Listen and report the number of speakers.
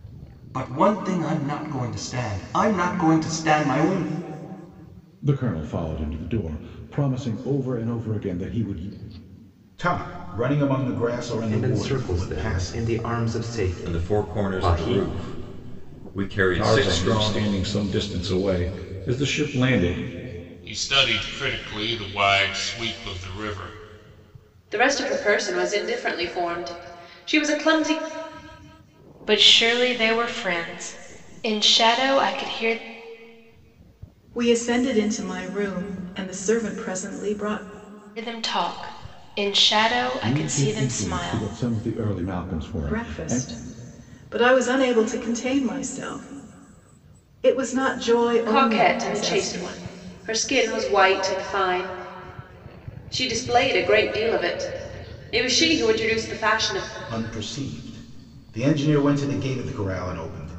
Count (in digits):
10